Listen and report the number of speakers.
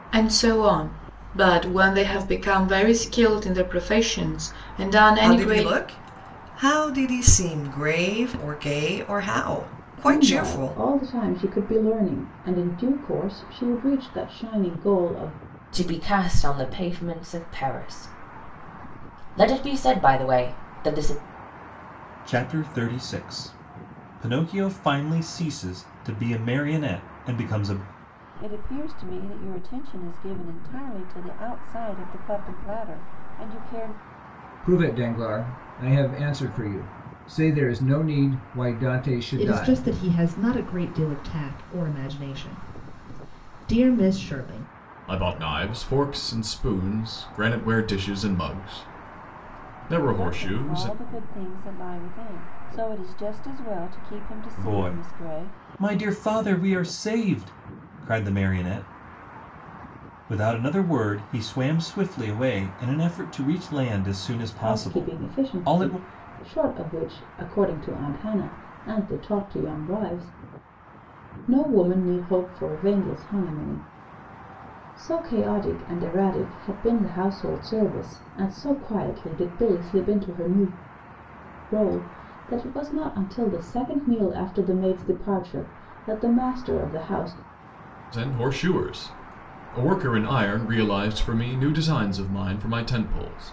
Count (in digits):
9